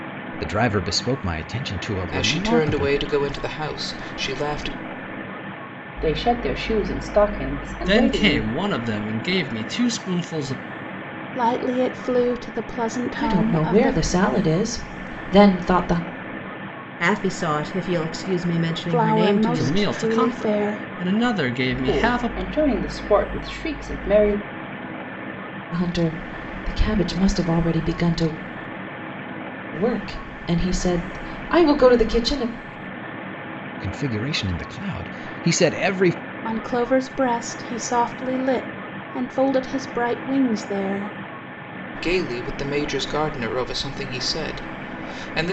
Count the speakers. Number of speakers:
seven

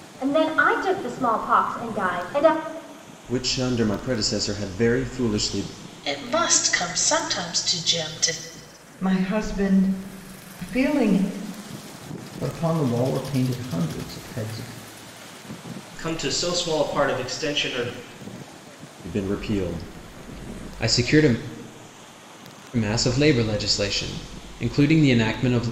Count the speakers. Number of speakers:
six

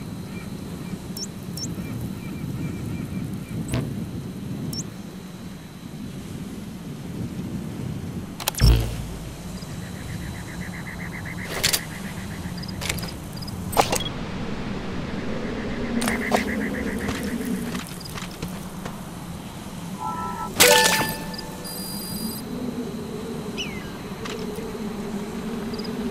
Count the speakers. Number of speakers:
zero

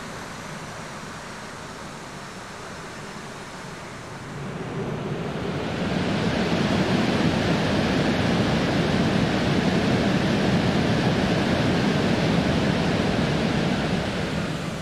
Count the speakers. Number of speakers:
zero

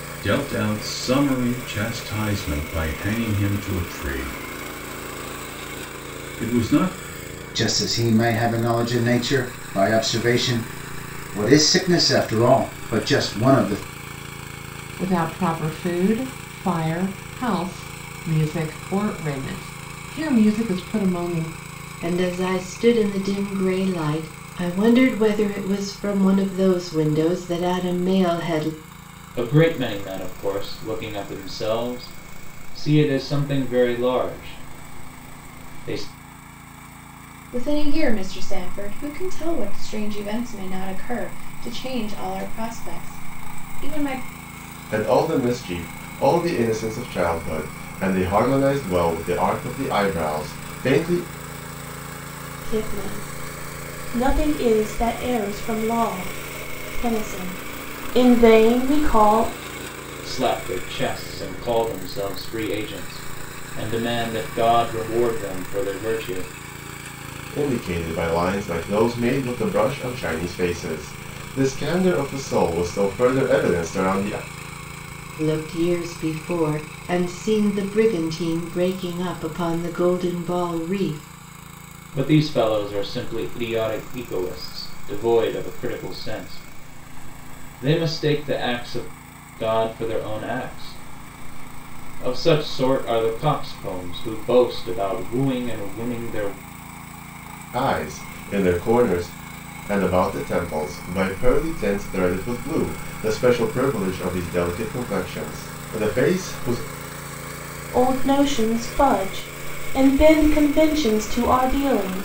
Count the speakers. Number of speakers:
eight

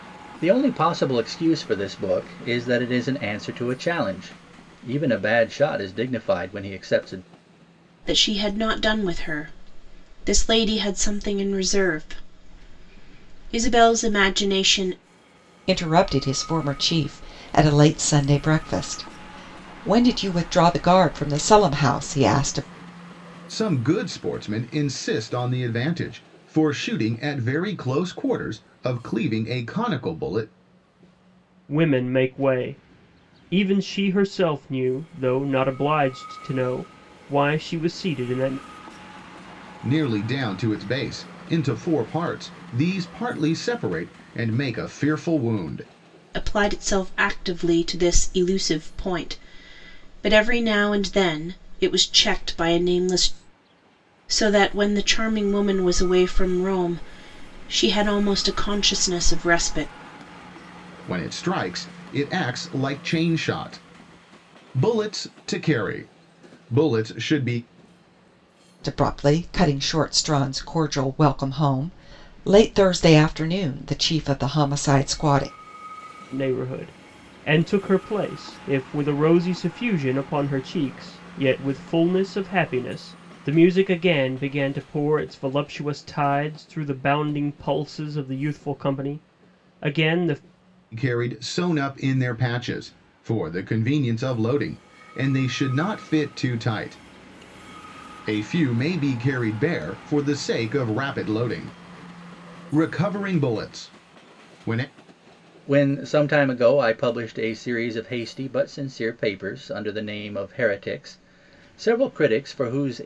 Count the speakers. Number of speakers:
five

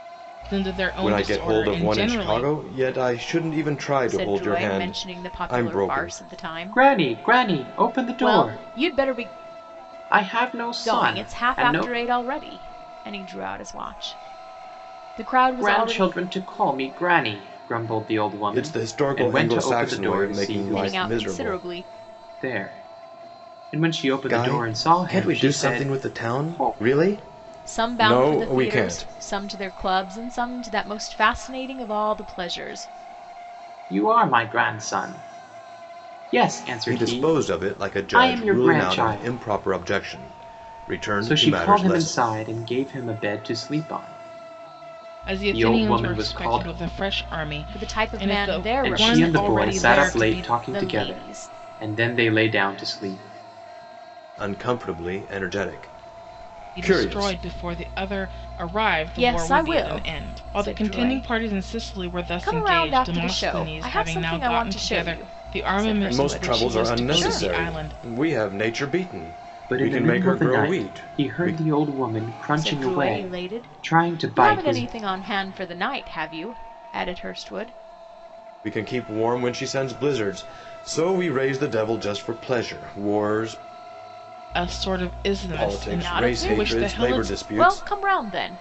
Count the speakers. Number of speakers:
four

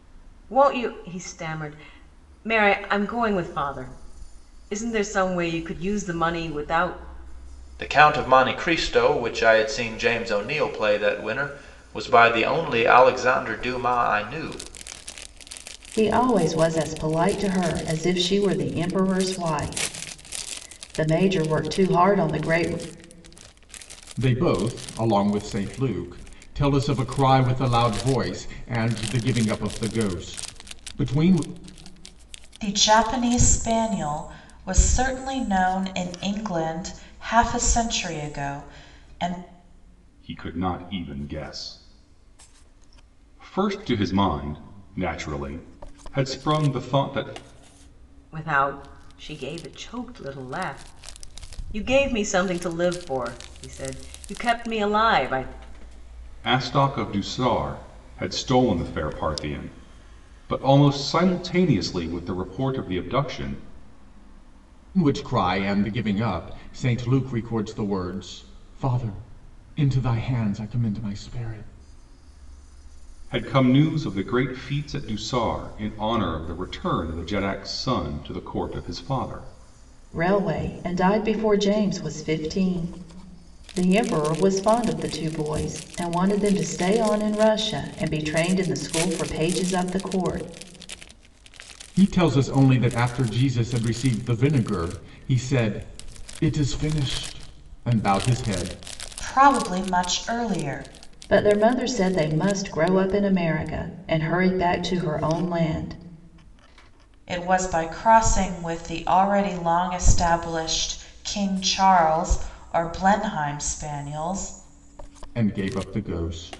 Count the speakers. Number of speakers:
six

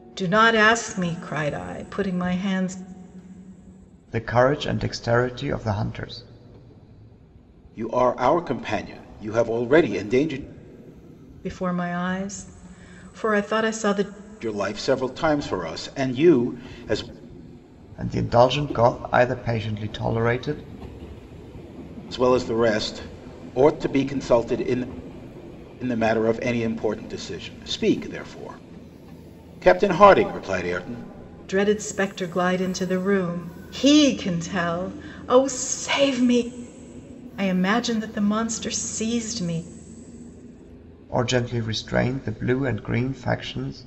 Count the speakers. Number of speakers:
three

